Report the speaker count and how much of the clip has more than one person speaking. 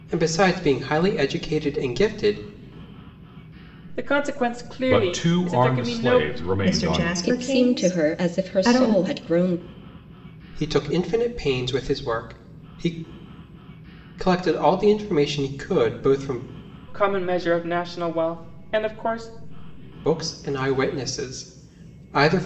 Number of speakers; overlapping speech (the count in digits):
5, about 16%